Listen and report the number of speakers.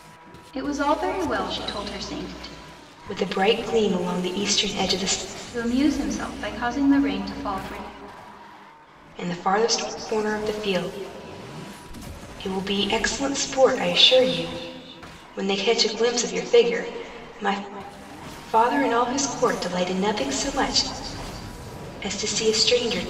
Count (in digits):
2